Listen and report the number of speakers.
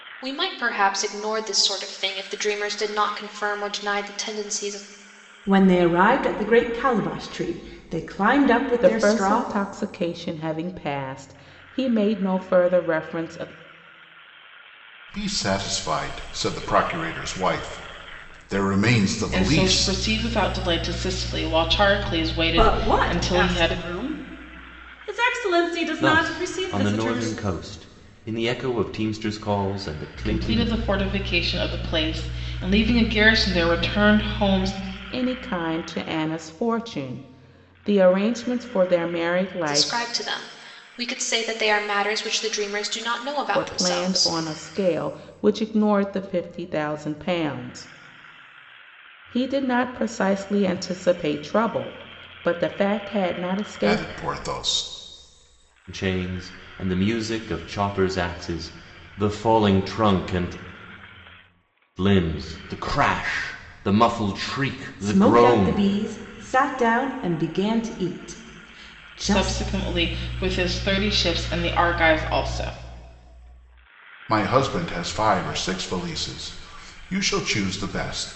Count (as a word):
seven